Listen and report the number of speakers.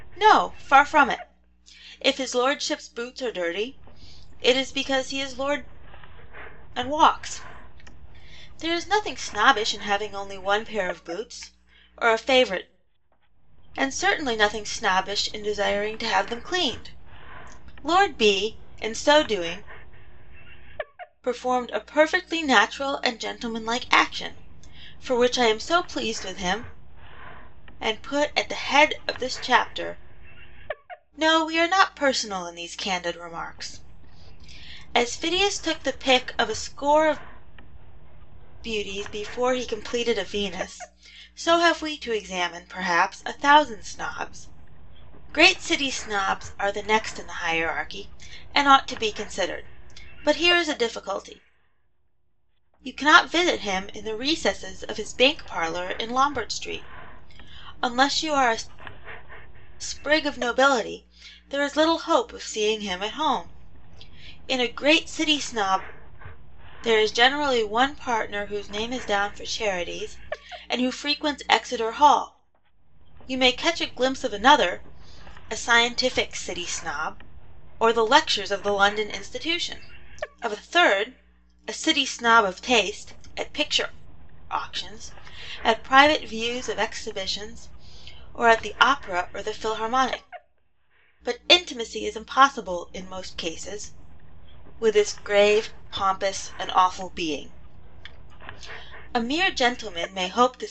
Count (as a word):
one